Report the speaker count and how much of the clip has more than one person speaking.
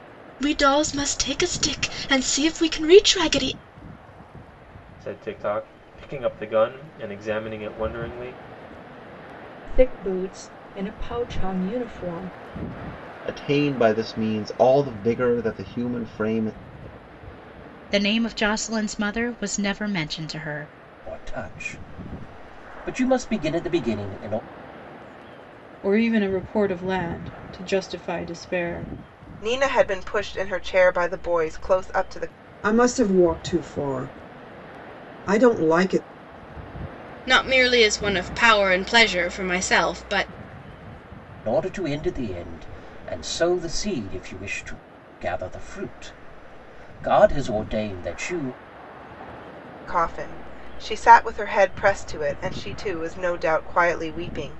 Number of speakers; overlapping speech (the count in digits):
10, no overlap